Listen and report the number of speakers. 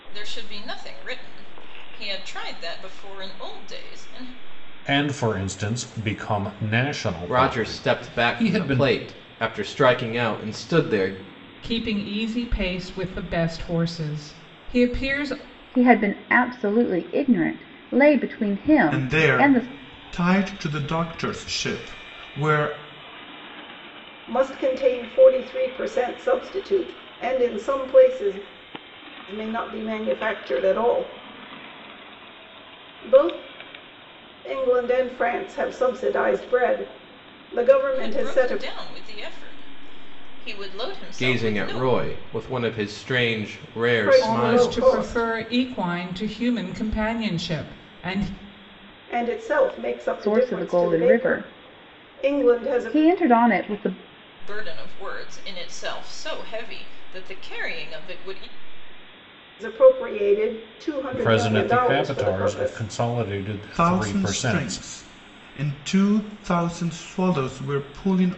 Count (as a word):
seven